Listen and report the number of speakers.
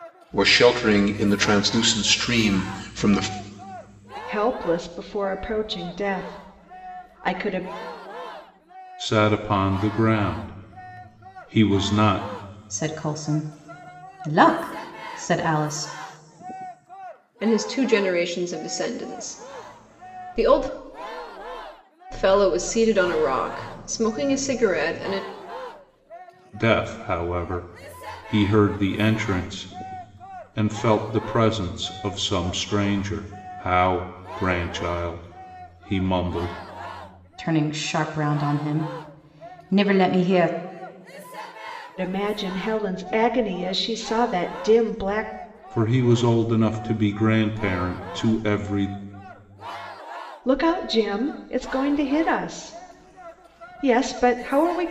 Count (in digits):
5